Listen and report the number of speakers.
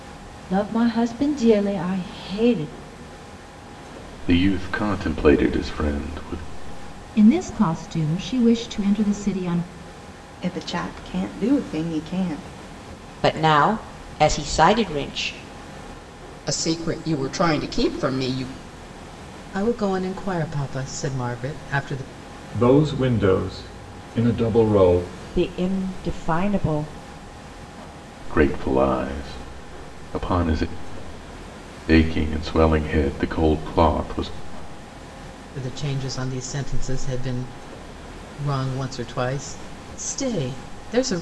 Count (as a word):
nine